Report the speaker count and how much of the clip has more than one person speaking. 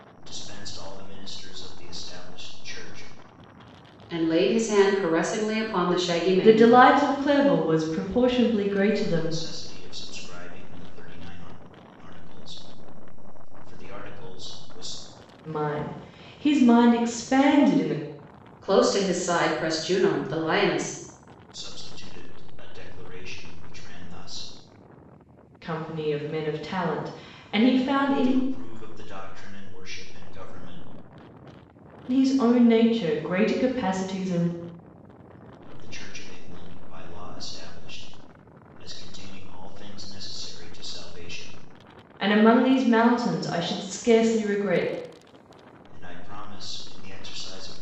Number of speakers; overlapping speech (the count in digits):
3, about 2%